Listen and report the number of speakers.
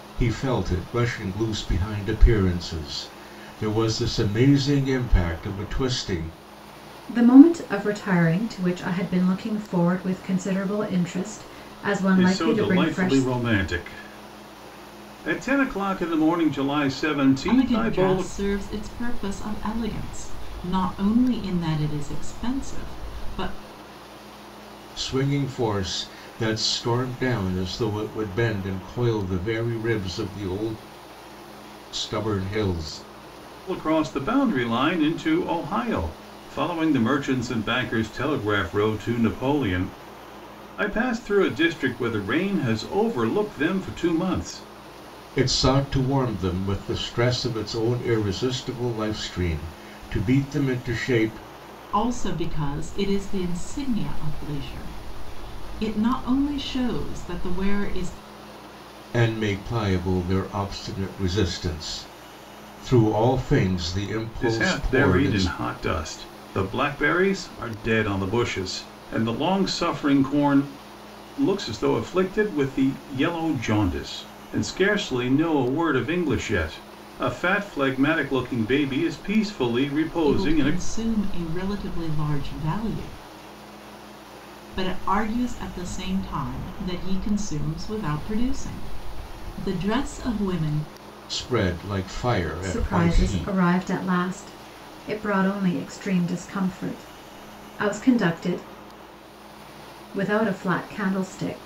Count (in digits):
4